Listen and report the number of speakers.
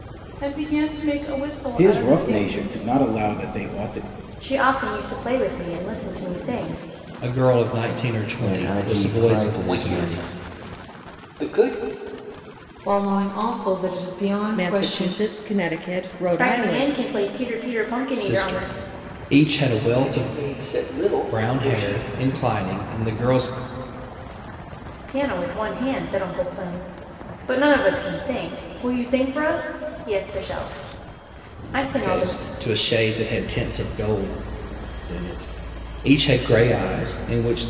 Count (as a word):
eight